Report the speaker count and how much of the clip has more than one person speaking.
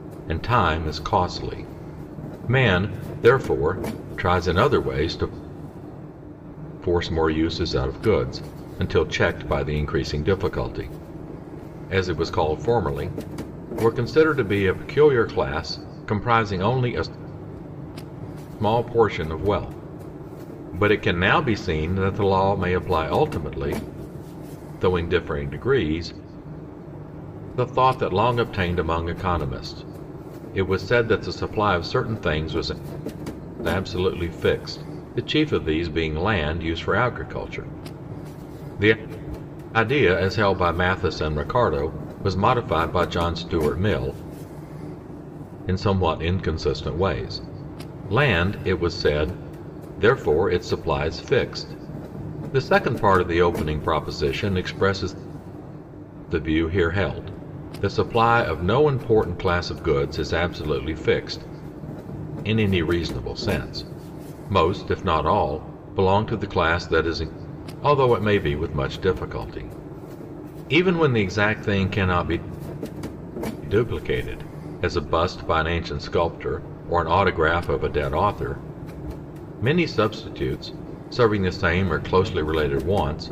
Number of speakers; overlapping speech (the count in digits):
1, no overlap